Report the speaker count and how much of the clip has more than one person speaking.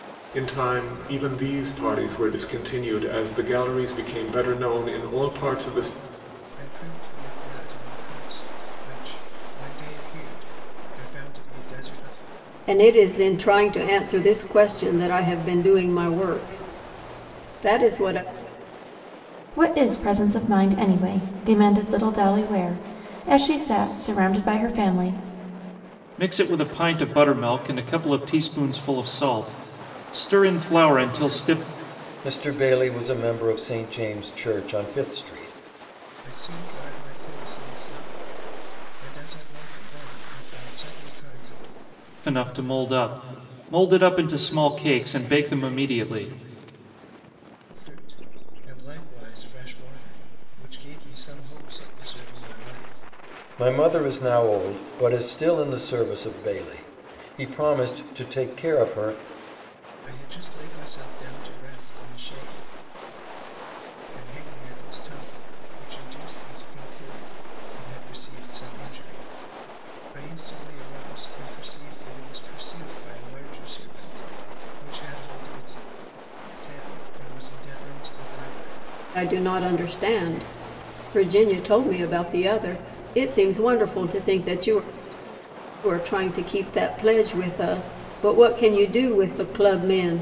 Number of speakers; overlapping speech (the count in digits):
6, no overlap